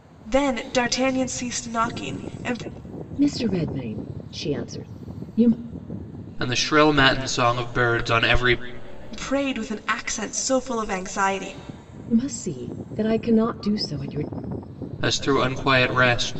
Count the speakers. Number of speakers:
3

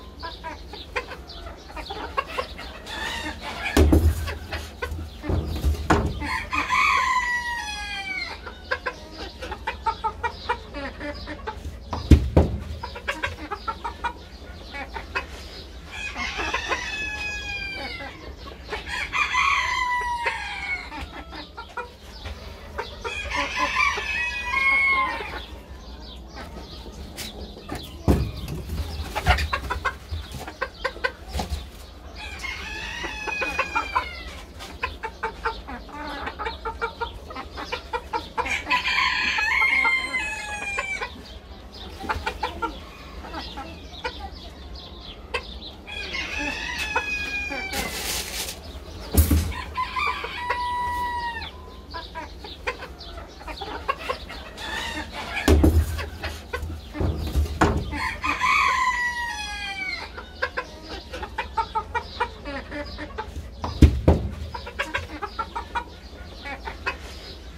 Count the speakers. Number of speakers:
0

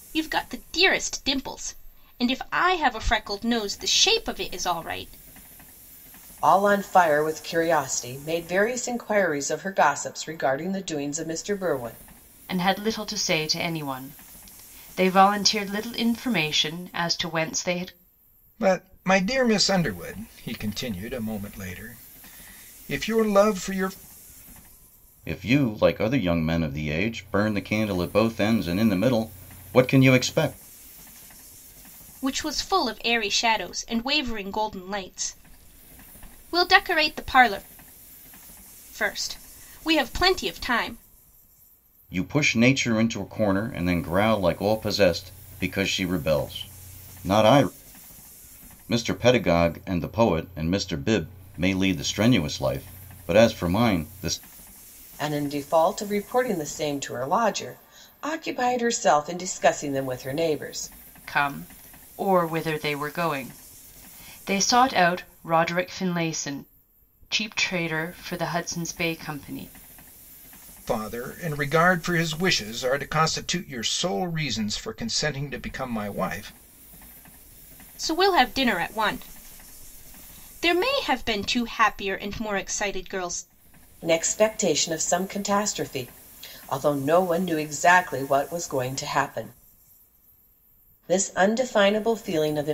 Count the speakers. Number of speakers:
5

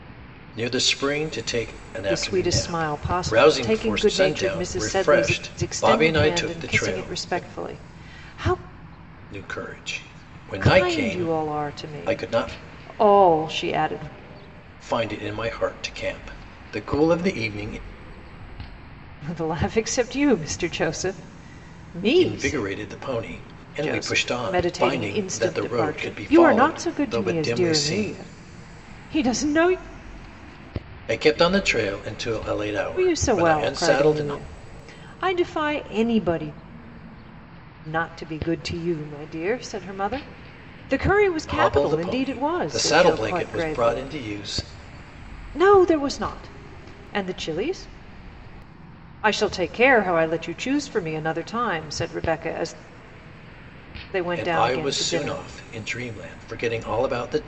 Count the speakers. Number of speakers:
2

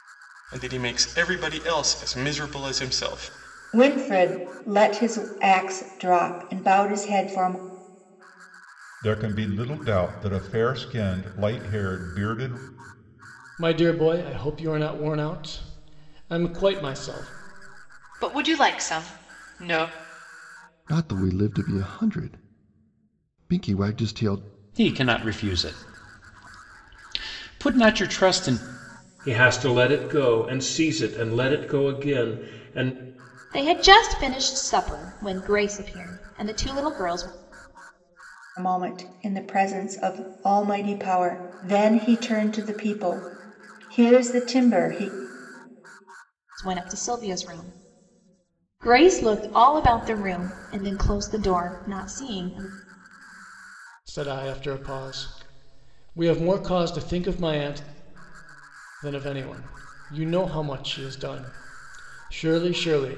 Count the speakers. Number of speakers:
9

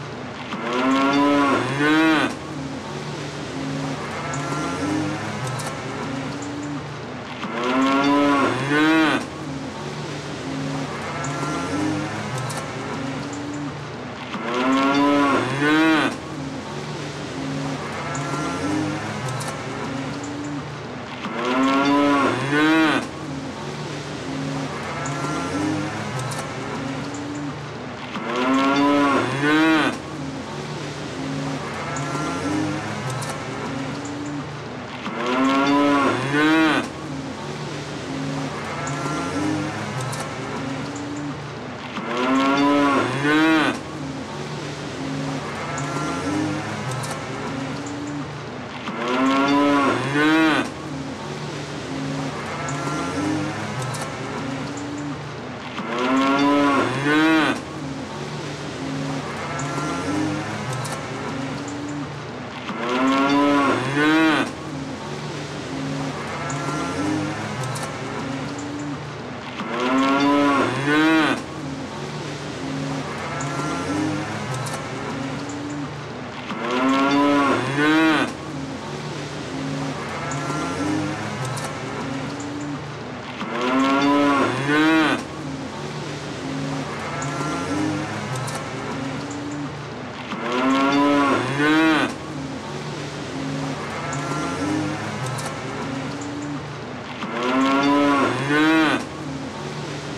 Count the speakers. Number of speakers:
0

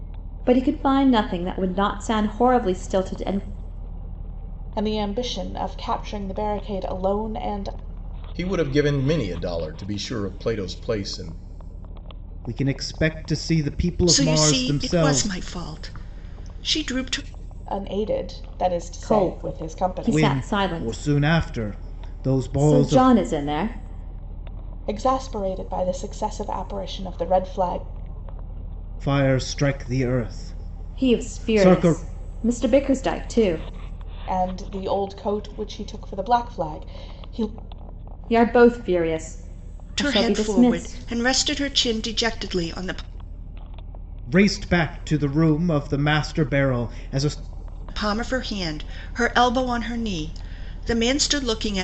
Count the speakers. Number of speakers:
5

